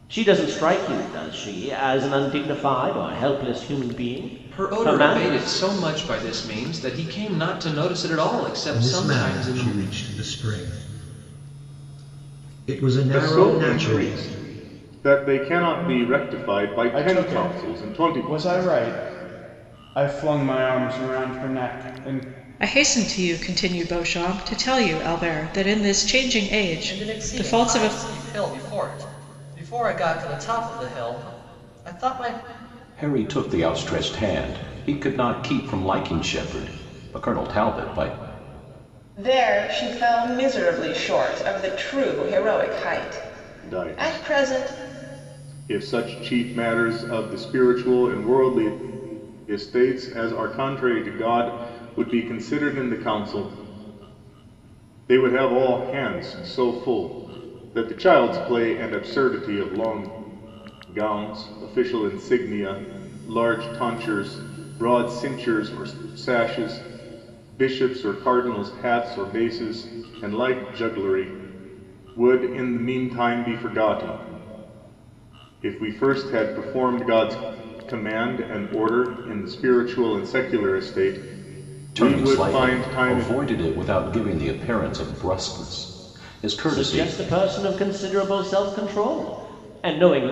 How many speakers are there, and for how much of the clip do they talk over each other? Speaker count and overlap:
9, about 10%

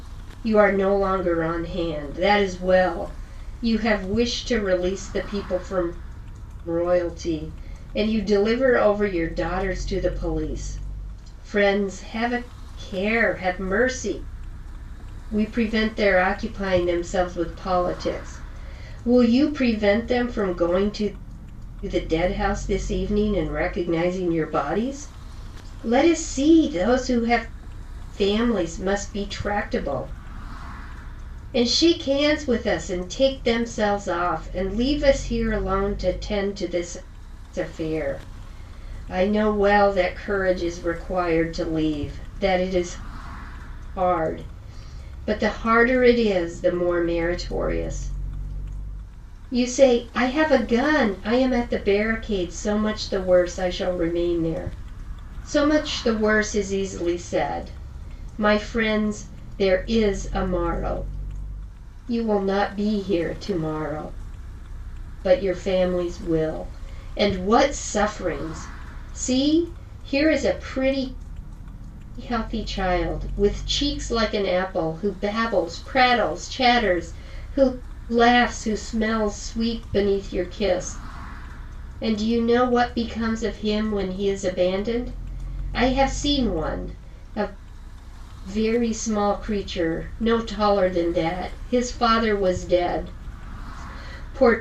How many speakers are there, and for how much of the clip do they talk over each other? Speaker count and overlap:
1, no overlap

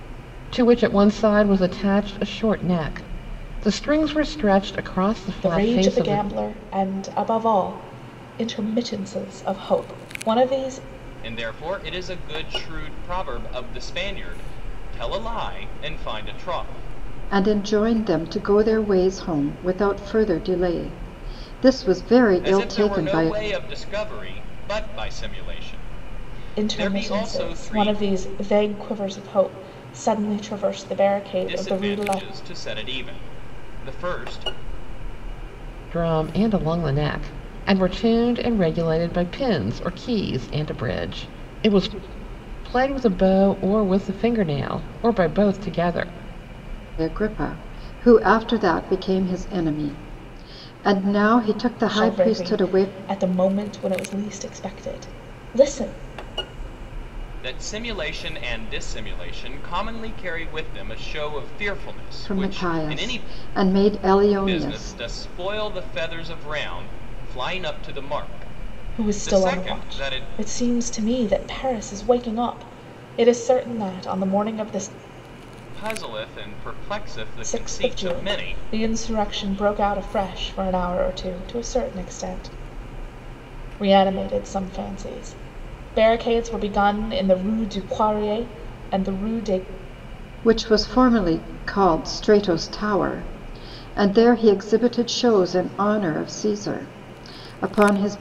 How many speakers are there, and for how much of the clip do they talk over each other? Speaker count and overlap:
4, about 10%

